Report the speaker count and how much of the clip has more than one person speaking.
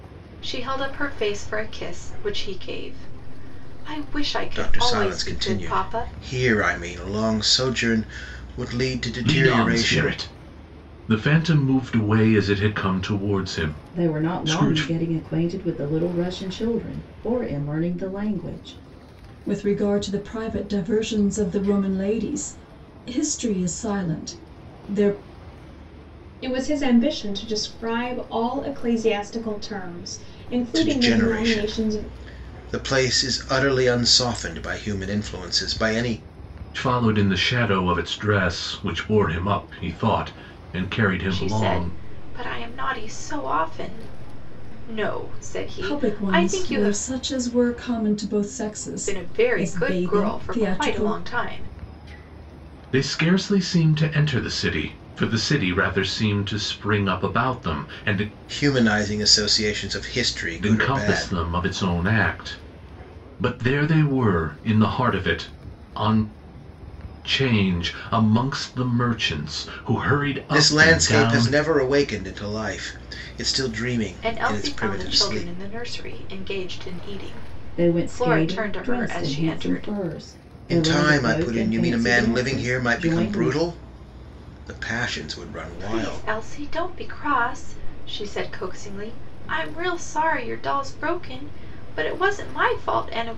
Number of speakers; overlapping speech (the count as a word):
six, about 19%